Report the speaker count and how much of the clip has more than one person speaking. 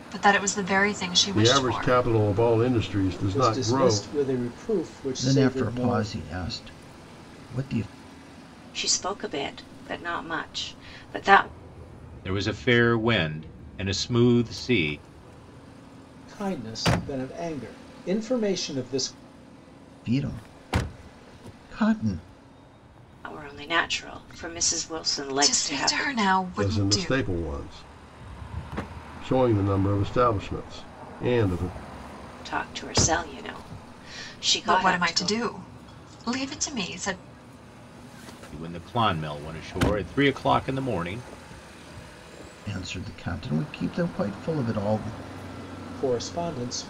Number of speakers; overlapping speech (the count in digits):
6, about 10%